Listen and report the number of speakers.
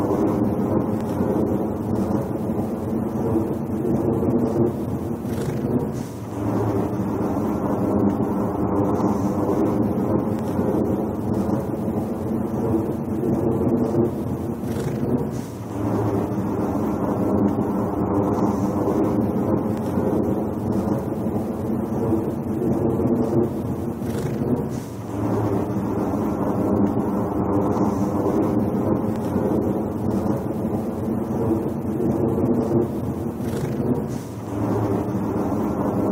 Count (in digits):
0